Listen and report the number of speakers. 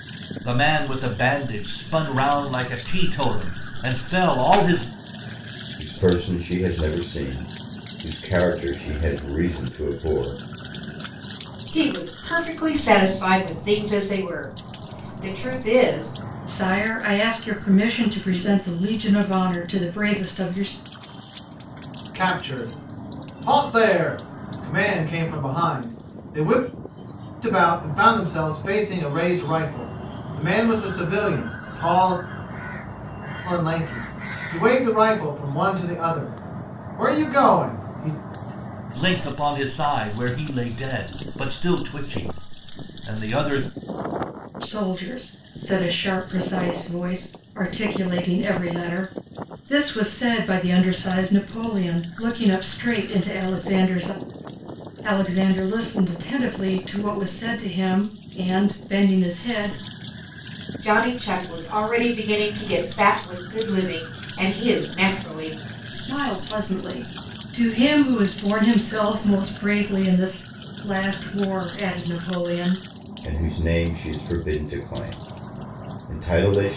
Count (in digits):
5